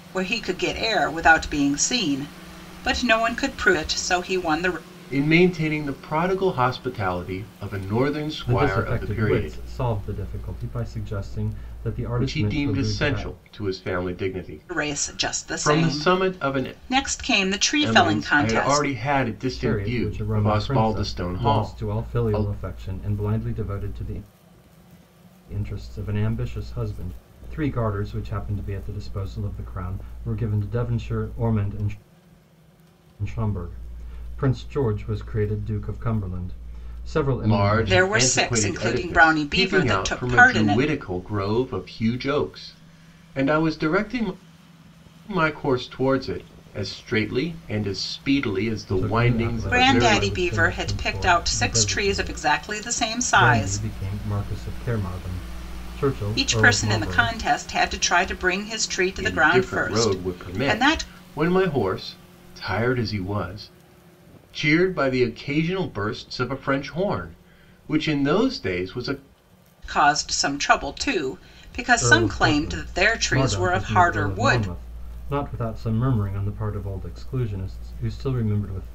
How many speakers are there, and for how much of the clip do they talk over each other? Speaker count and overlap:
three, about 28%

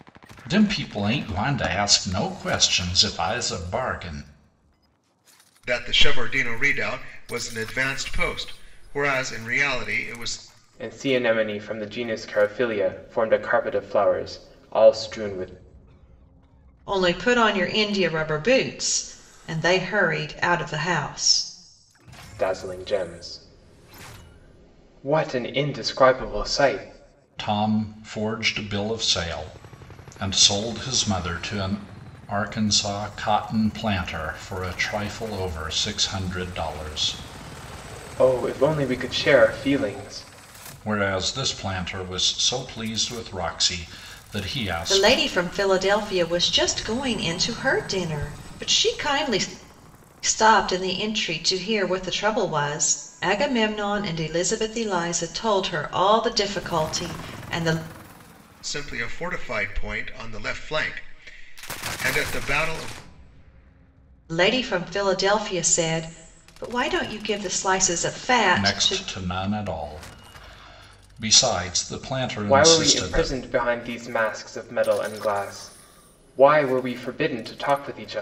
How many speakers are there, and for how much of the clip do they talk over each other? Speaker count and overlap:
four, about 2%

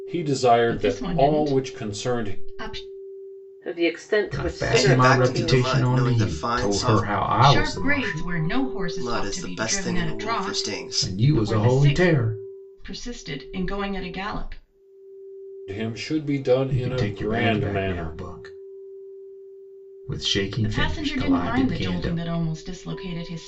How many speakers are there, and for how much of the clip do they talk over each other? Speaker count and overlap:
five, about 50%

